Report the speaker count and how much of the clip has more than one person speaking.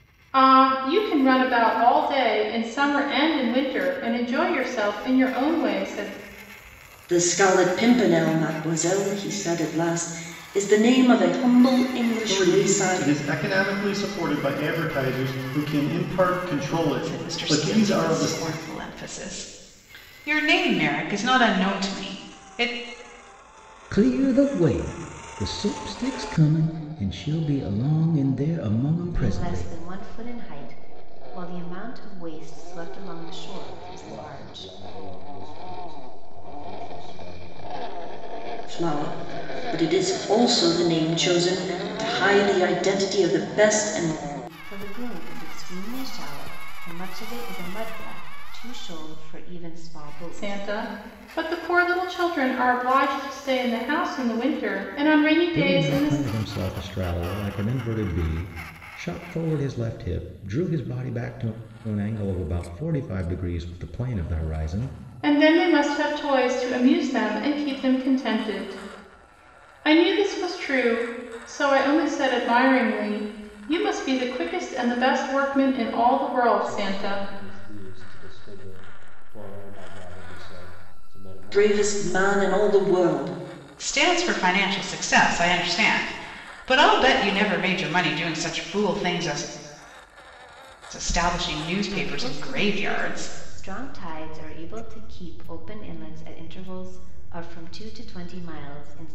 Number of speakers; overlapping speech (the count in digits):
7, about 10%